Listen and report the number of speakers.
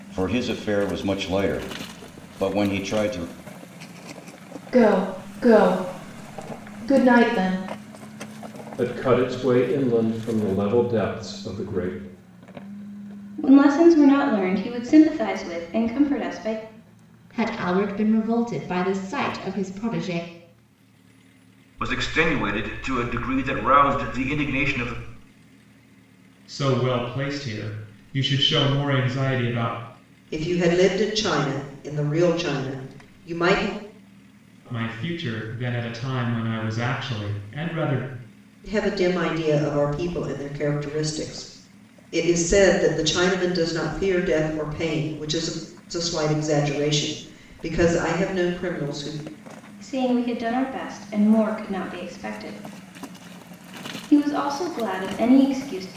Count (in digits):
8